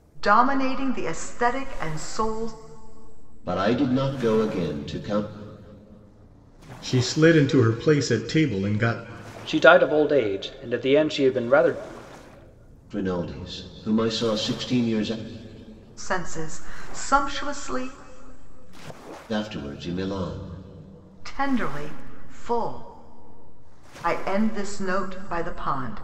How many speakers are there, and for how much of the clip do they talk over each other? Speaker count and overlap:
4, no overlap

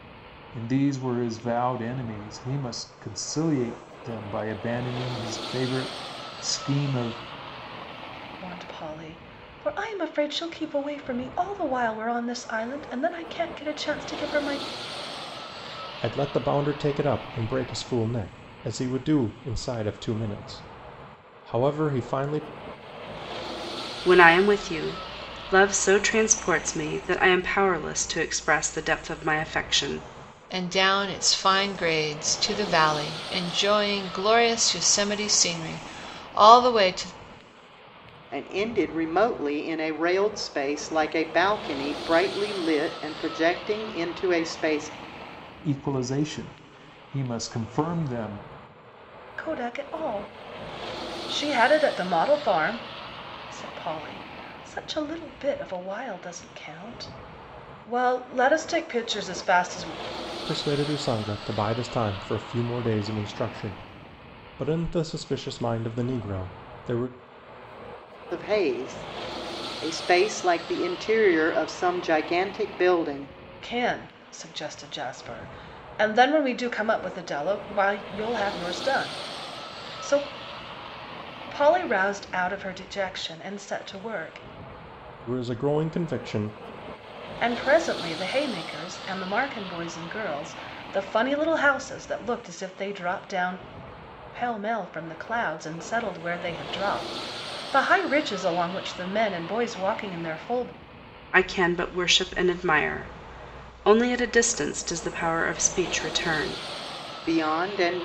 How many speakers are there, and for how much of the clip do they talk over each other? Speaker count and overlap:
6, no overlap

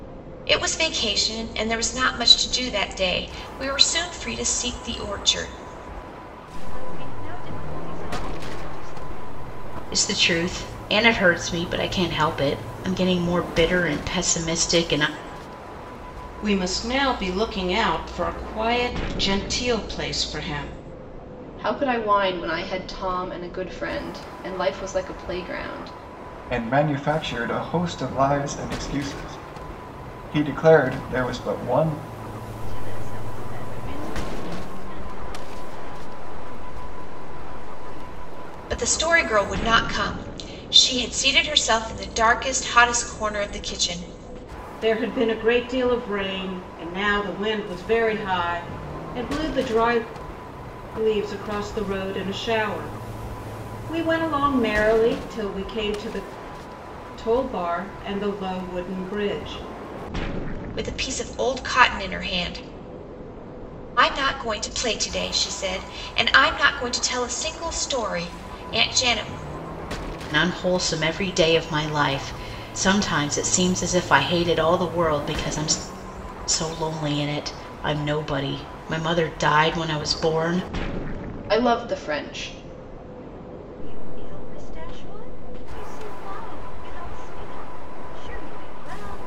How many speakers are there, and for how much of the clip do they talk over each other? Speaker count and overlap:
6, no overlap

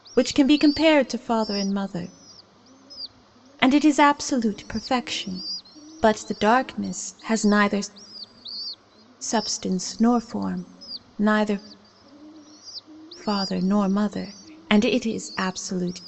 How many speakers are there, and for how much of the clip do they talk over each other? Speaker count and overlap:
1, no overlap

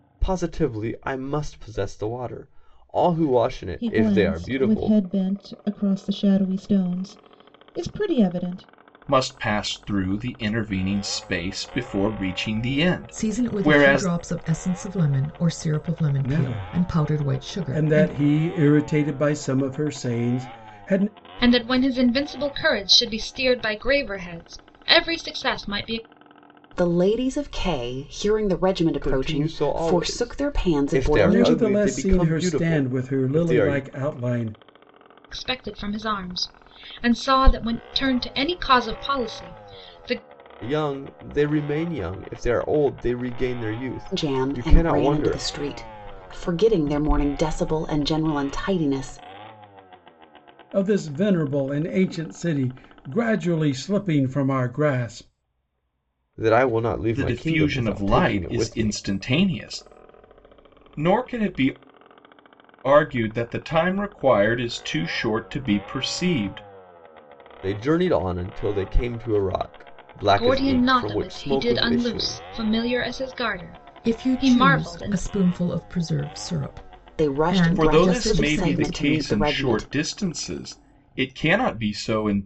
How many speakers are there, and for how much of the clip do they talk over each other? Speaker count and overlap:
7, about 22%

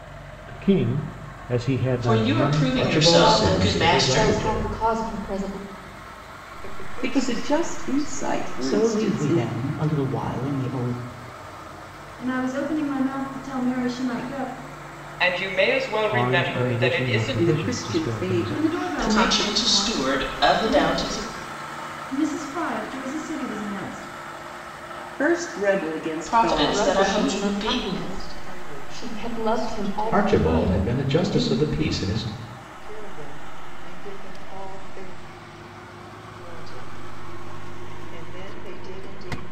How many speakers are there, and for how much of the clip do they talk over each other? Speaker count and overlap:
9, about 38%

